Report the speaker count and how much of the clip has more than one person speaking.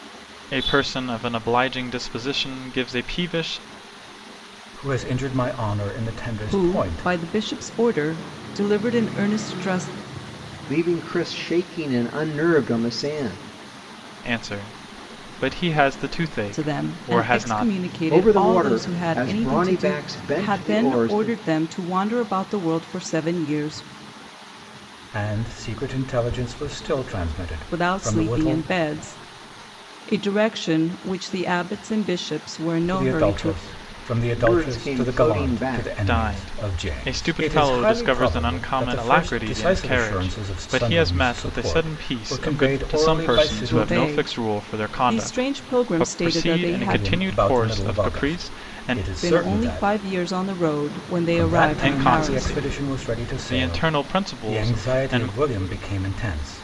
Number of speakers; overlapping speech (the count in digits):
4, about 45%